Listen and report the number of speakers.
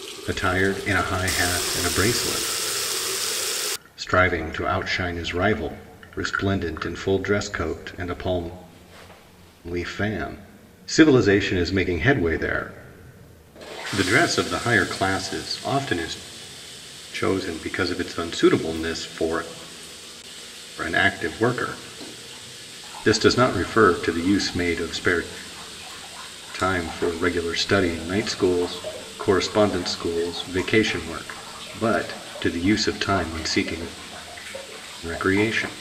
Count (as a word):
one